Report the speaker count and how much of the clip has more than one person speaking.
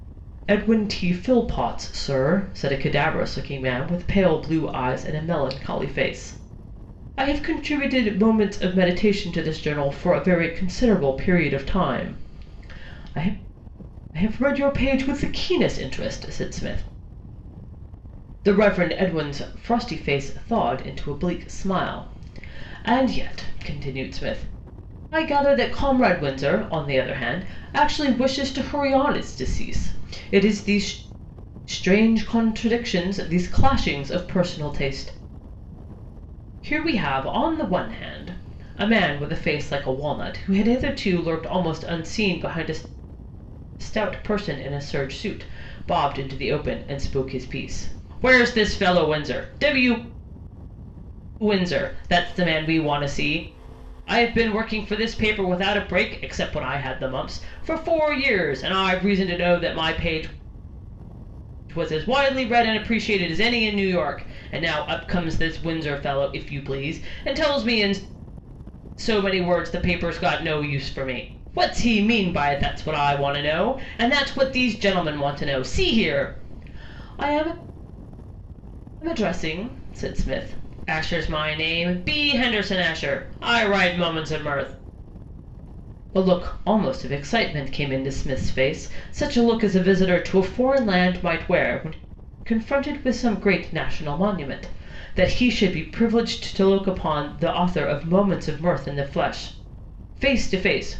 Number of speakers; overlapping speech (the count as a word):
one, no overlap